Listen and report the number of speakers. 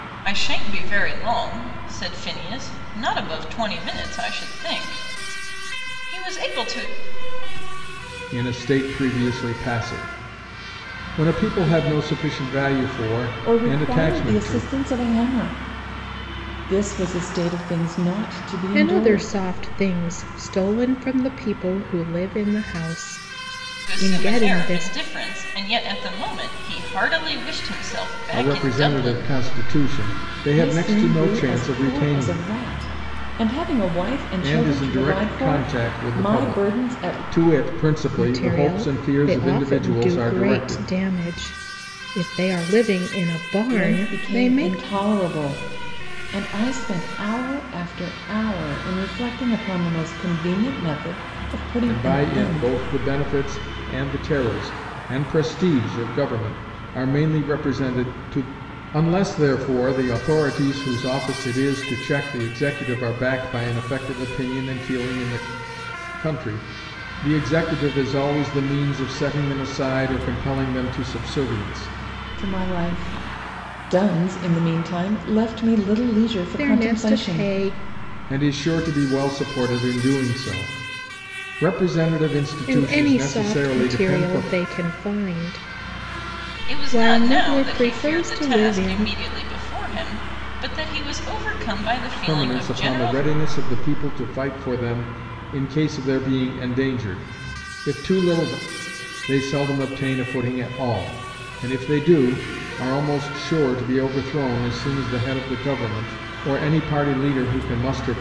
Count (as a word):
four